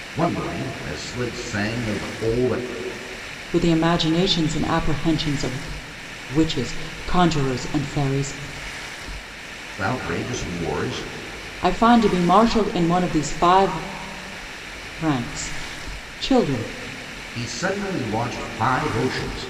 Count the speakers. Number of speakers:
2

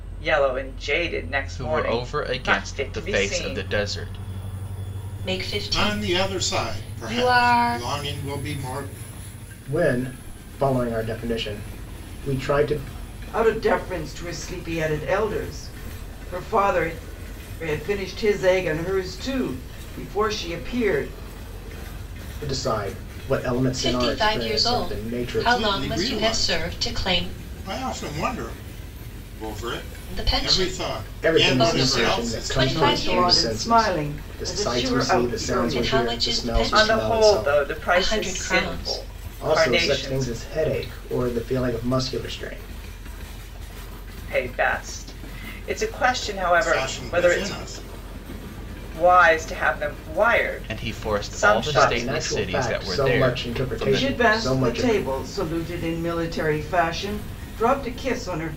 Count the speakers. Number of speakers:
6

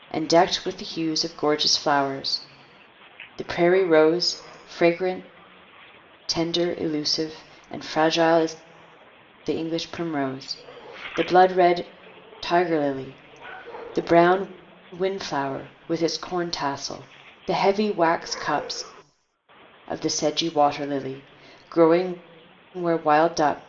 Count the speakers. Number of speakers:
1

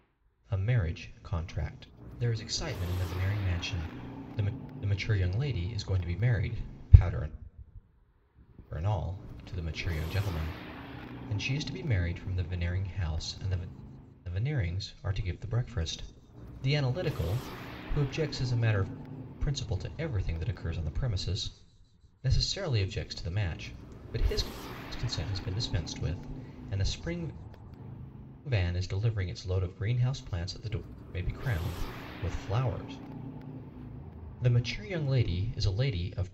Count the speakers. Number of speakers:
1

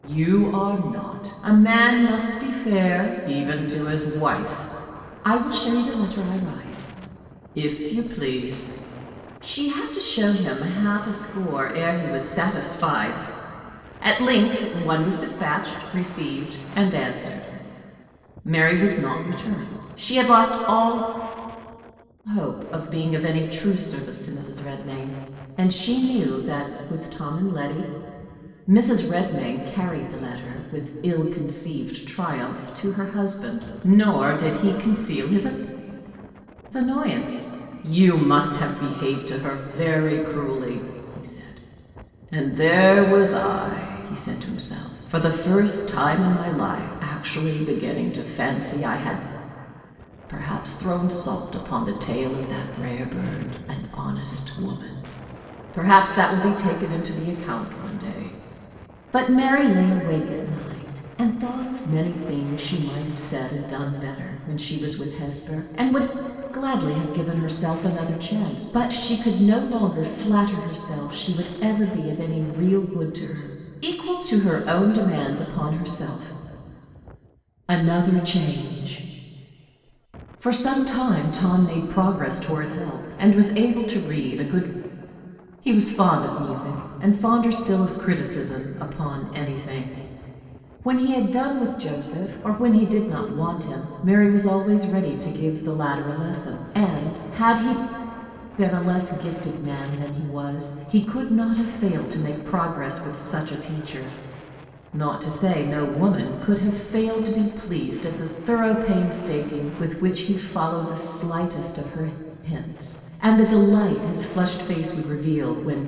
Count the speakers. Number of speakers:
1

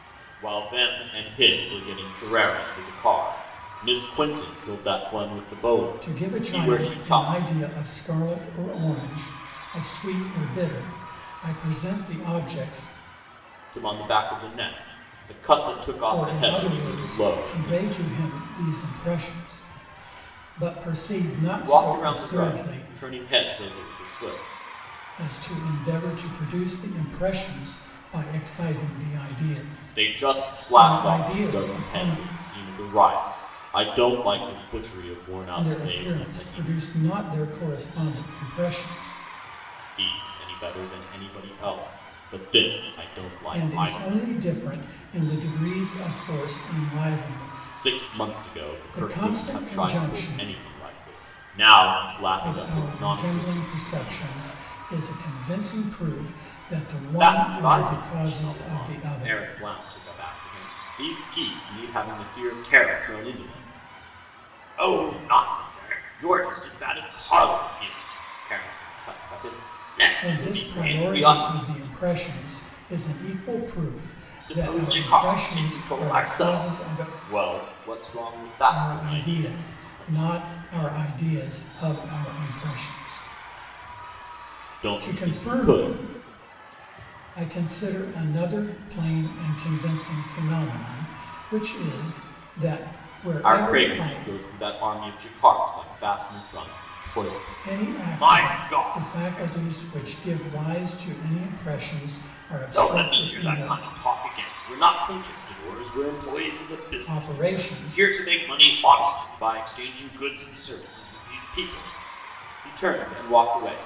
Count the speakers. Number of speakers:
2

